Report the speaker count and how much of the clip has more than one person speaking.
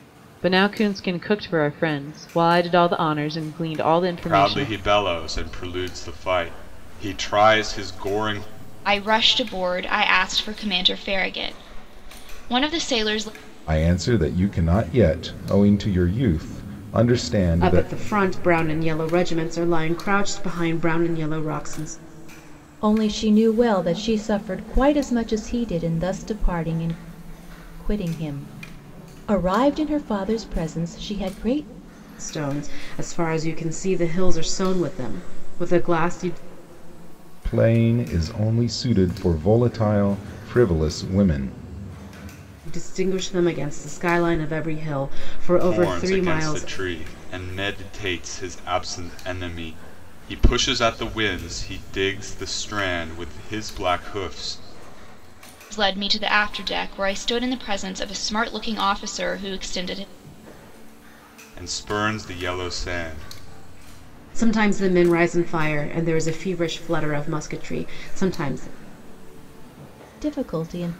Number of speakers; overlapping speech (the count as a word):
six, about 3%